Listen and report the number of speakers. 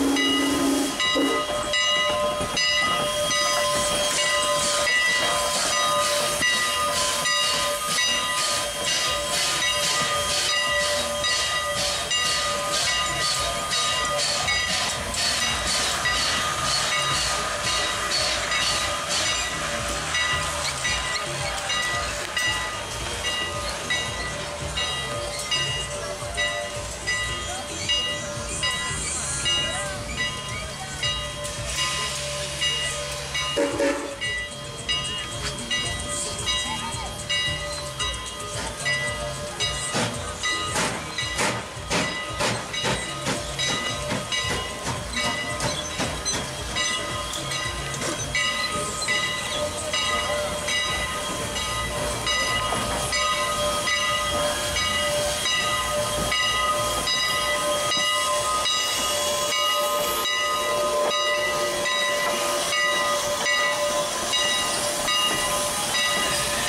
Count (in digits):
0